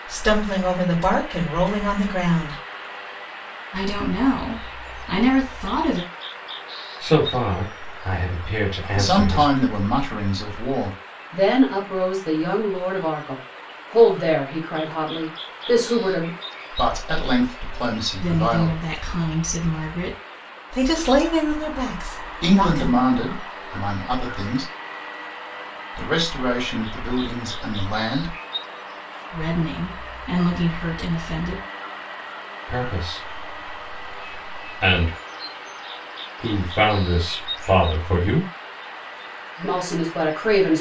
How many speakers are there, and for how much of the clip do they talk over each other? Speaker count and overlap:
five, about 5%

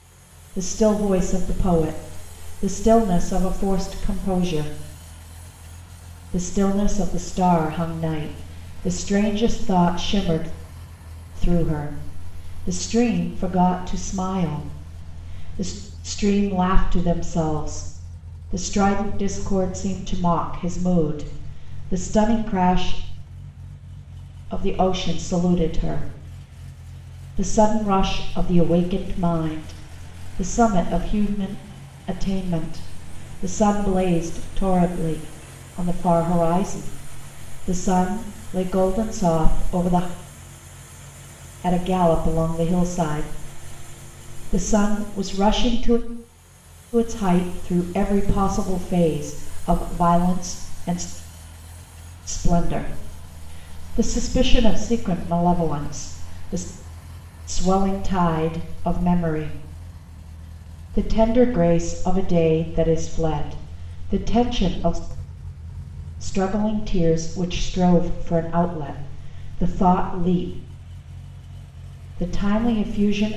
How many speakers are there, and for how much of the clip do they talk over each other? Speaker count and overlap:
one, no overlap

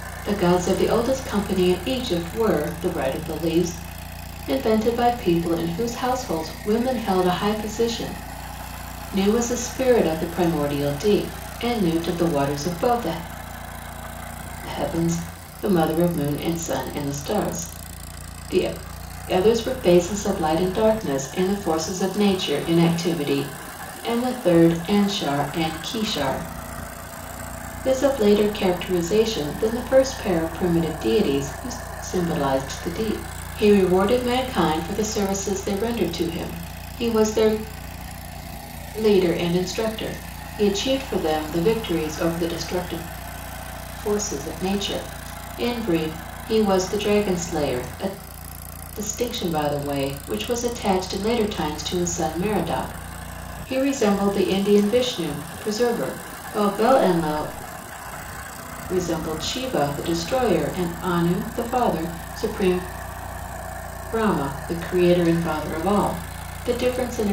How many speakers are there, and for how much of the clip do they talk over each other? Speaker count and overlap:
one, no overlap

